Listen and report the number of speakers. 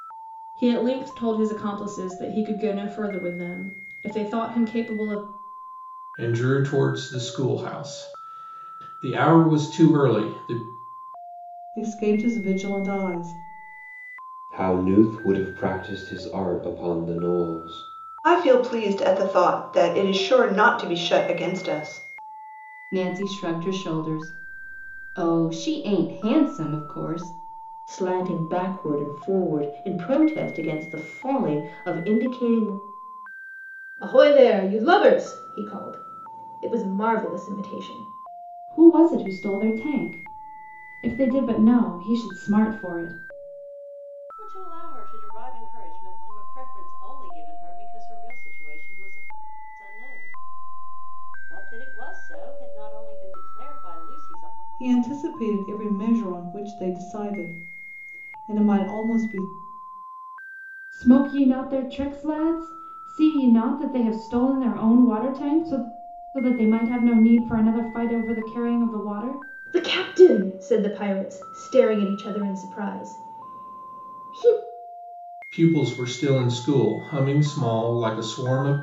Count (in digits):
10